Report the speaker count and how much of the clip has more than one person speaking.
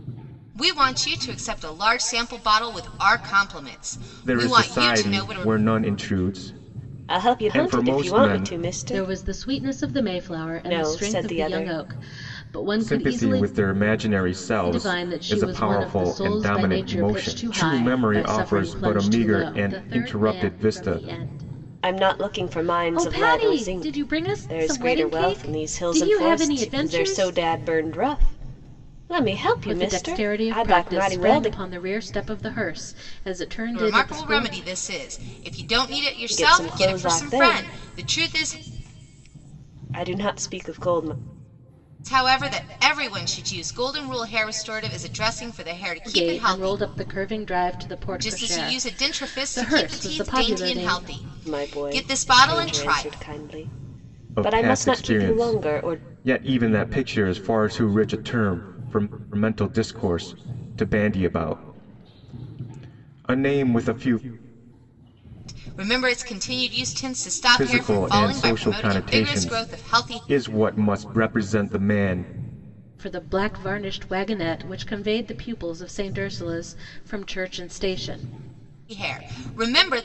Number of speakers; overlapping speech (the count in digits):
4, about 41%